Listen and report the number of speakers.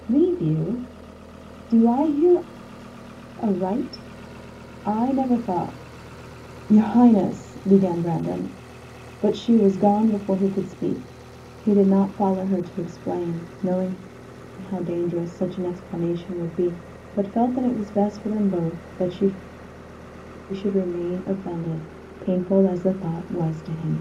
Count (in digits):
1